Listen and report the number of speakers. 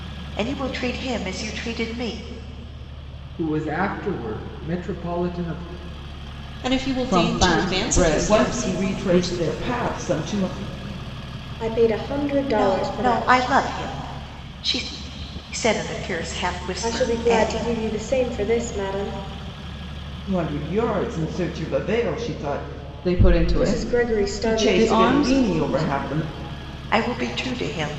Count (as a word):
six